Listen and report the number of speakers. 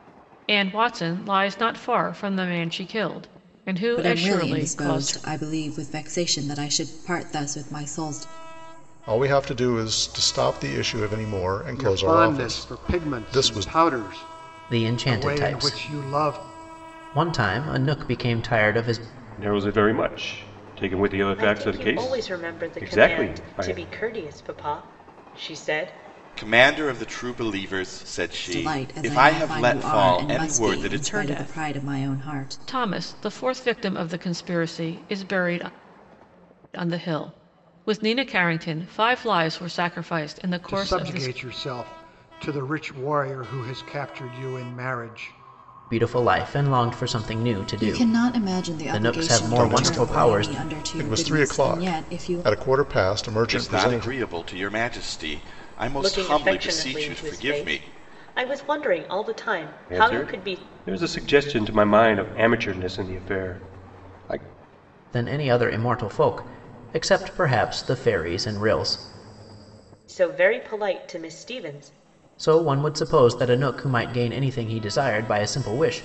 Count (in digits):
8